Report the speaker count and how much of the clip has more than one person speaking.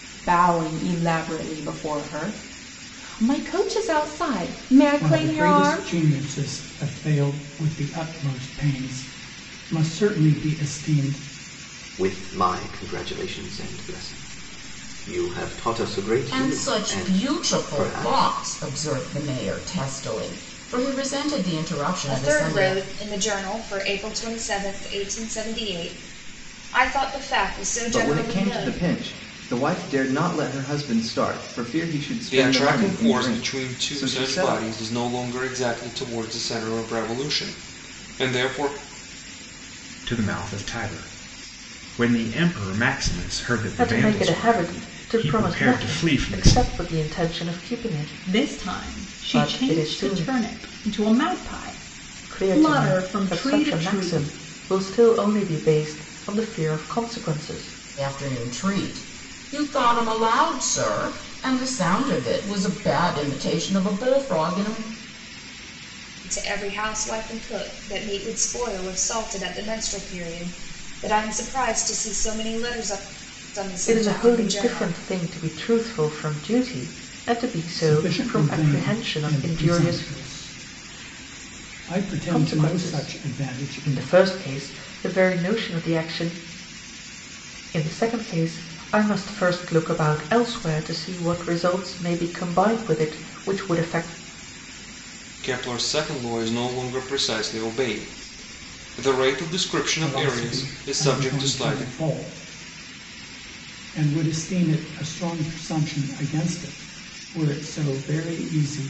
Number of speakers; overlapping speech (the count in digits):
10, about 20%